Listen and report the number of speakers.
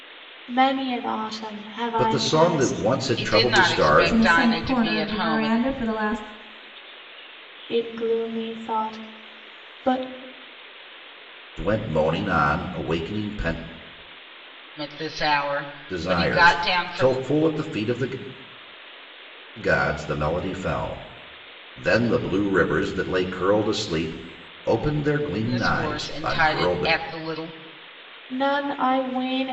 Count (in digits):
4